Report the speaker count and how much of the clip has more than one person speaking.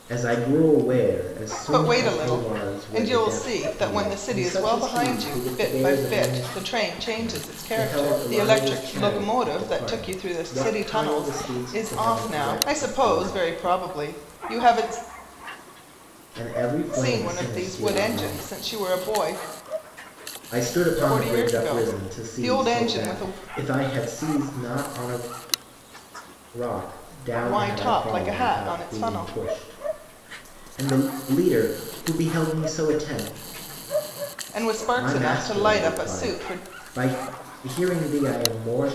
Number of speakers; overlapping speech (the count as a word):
two, about 49%